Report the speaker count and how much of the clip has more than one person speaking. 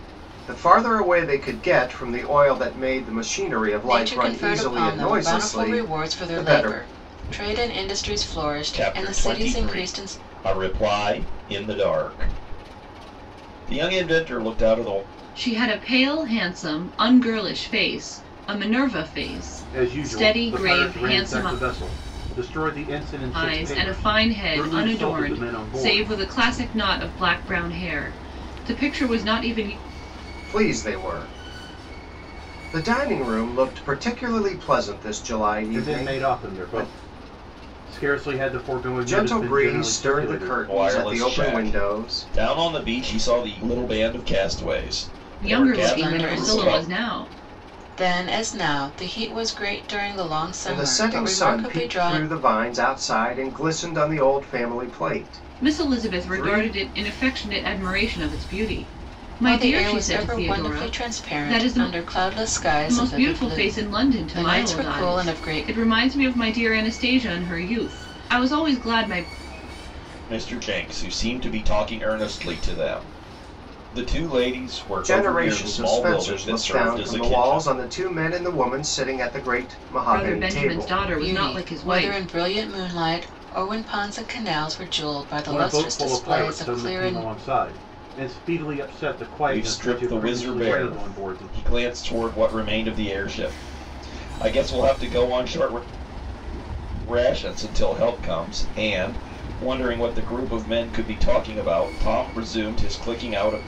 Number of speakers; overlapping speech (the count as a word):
five, about 31%